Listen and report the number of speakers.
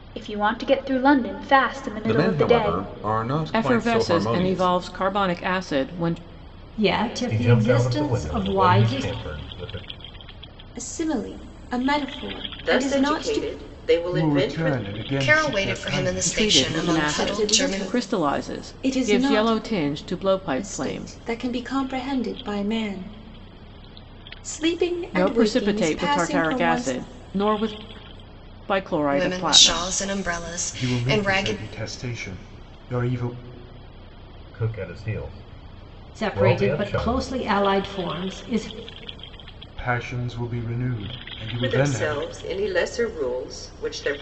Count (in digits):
9